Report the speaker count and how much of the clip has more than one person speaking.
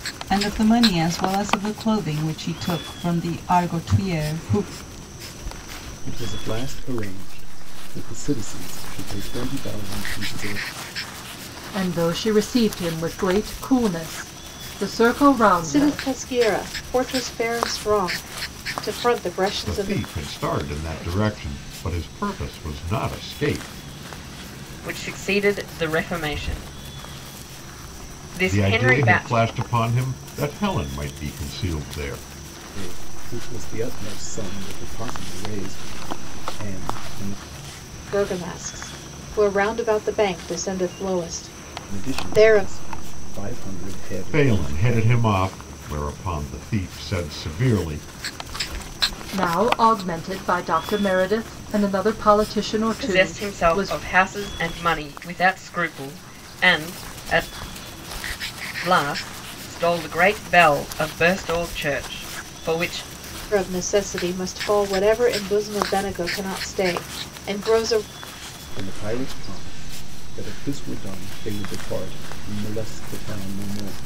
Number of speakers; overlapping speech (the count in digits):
6, about 6%